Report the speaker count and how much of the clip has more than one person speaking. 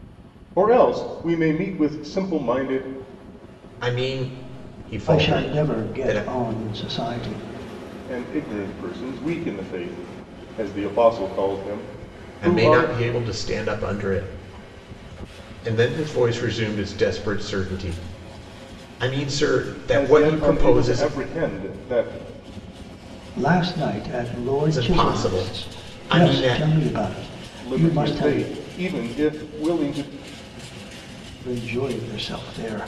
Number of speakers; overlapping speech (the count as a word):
three, about 16%